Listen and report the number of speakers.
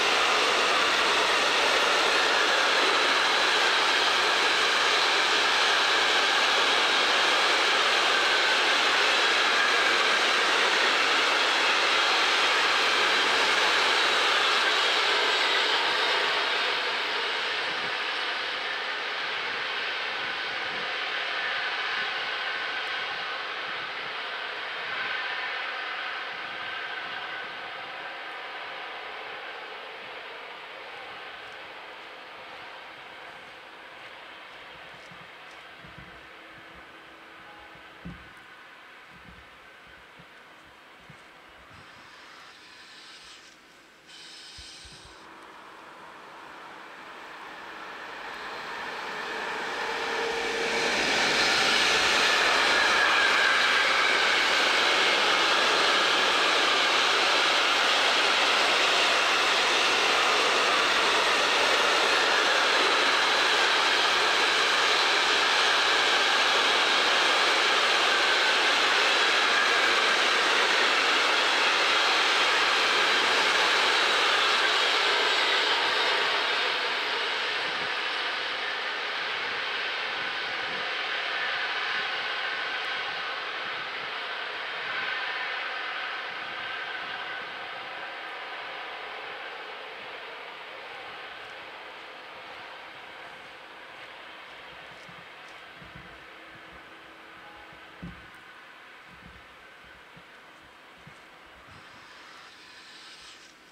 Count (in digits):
0